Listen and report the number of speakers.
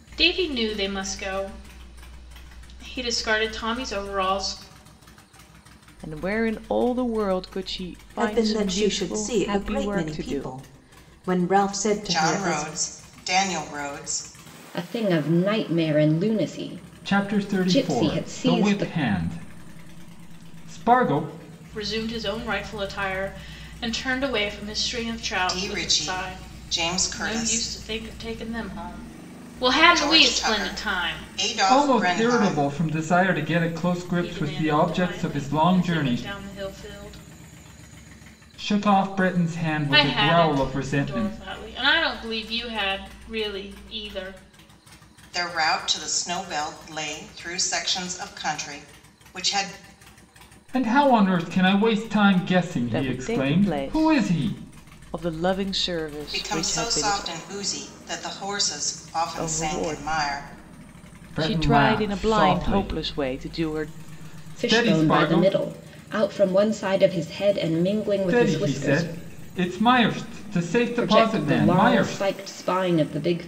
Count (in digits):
6